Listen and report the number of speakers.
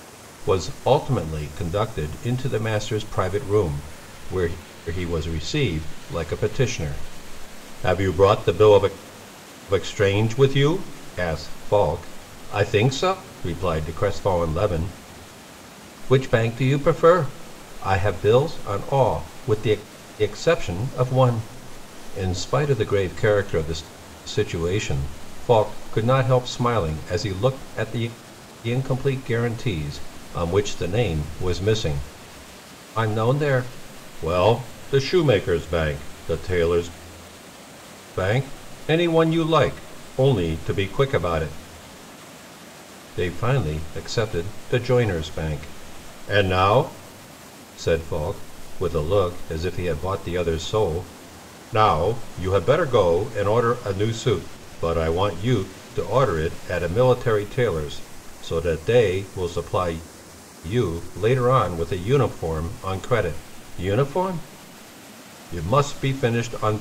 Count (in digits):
1